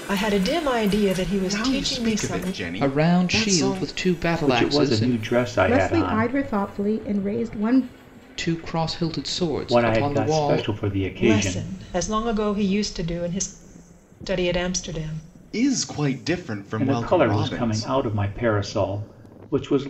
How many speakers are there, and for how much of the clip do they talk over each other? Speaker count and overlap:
five, about 32%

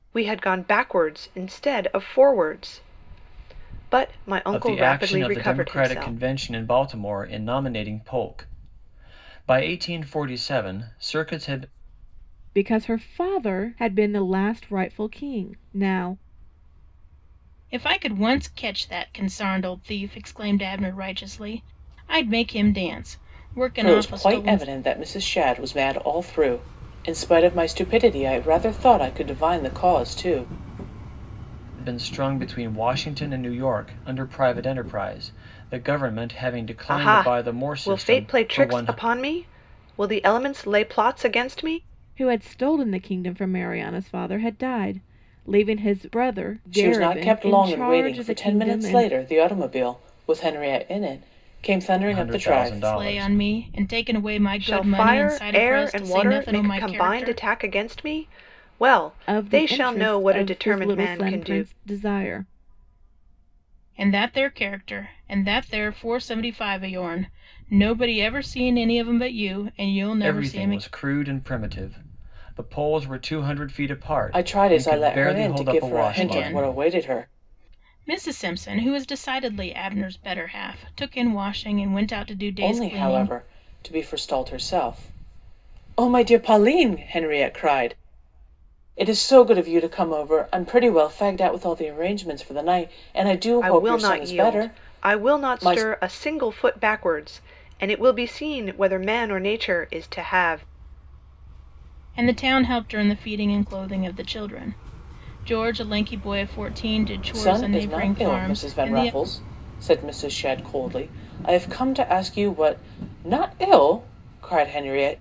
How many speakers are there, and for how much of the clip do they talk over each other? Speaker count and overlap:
five, about 19%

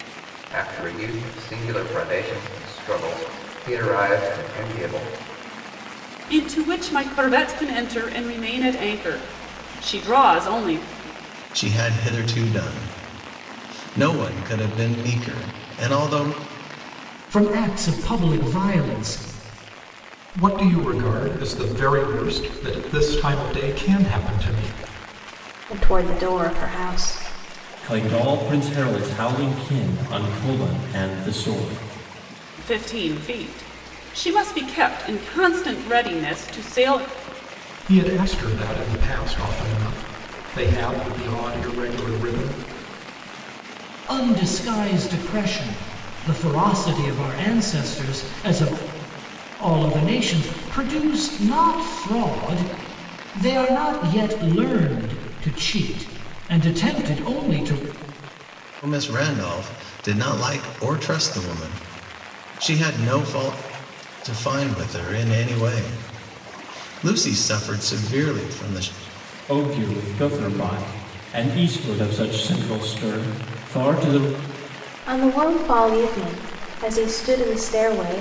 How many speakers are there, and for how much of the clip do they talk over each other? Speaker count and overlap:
seven, no overlap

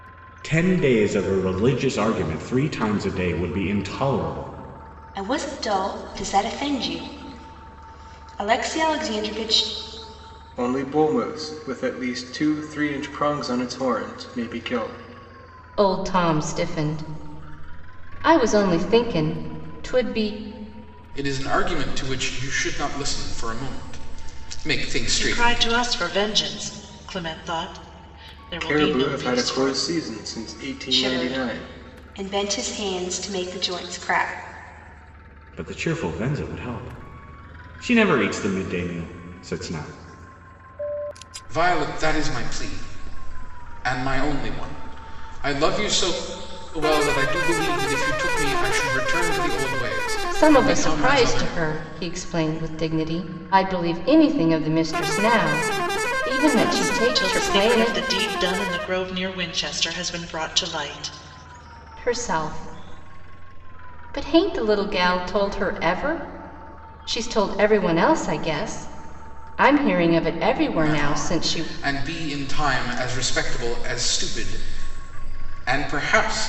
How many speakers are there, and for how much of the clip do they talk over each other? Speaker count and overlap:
six, about 8%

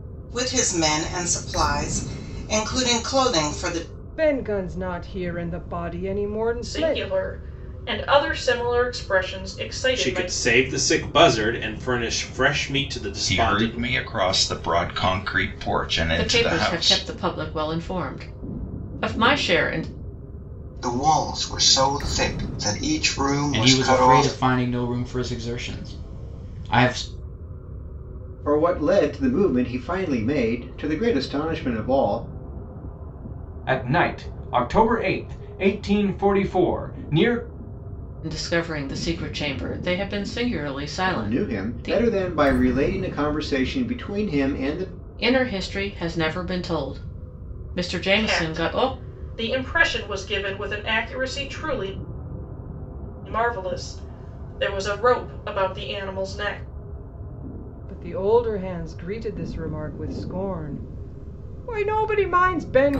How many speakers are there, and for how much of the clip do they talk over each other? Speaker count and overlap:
ten, about 8%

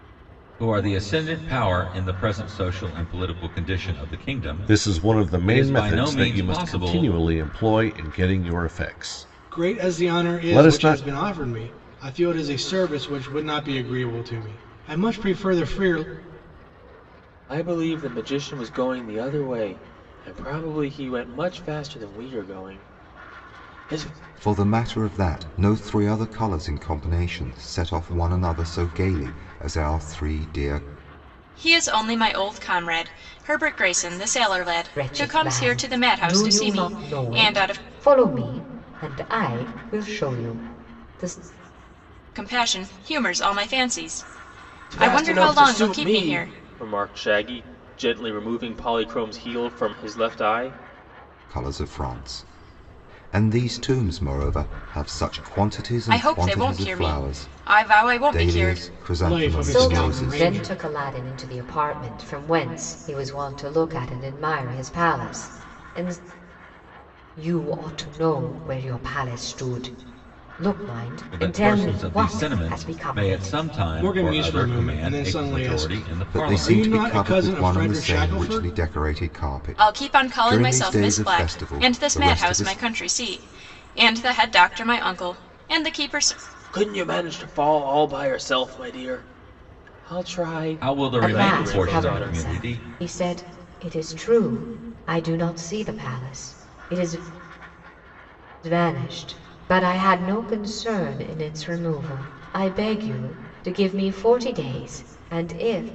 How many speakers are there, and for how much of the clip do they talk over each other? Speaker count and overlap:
seven, about 23%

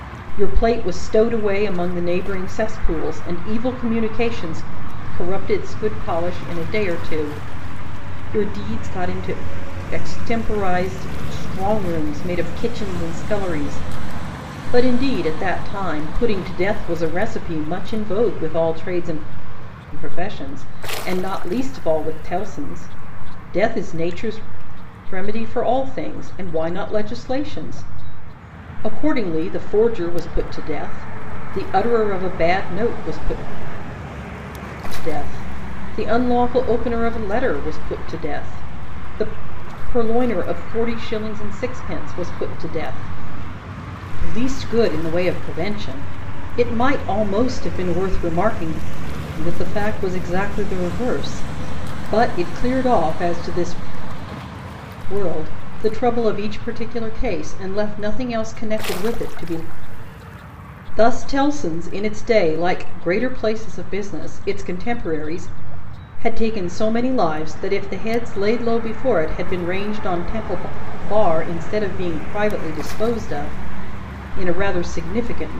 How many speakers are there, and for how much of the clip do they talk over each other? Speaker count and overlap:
one, no overlap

